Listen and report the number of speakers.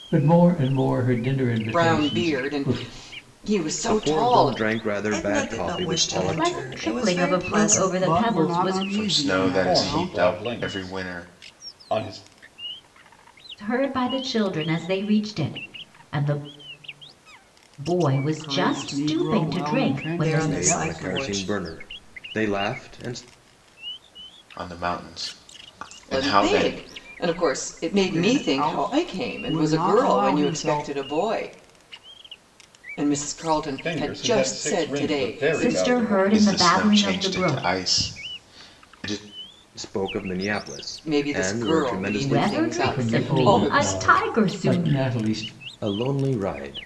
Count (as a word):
eight